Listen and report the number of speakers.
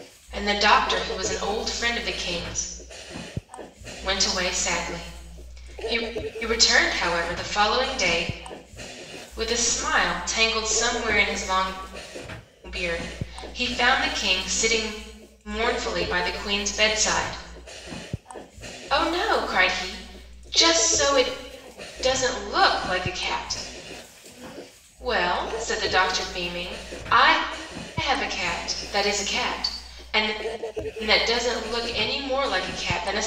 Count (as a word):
one